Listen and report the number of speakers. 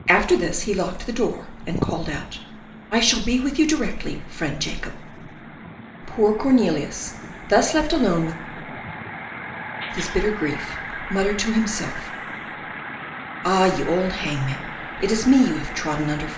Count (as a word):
one